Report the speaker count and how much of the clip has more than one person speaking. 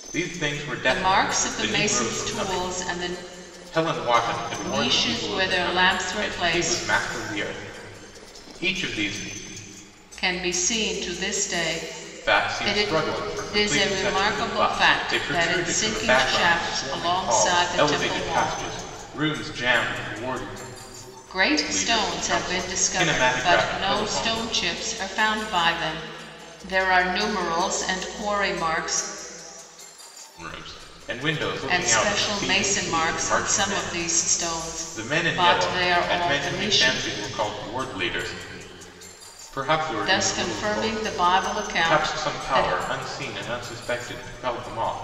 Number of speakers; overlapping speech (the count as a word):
two, about 46%